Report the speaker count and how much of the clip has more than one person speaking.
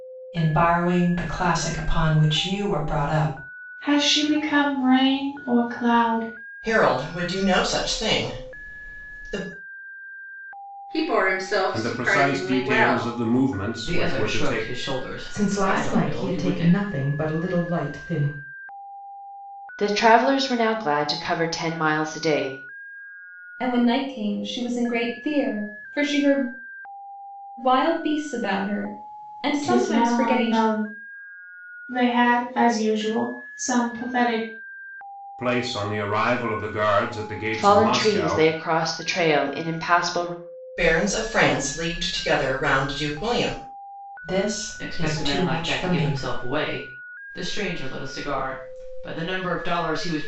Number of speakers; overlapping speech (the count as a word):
nine, about 14%